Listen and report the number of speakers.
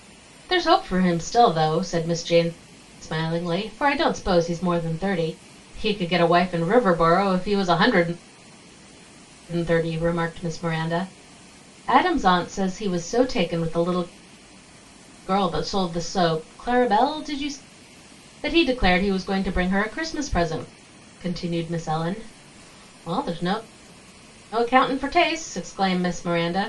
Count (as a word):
one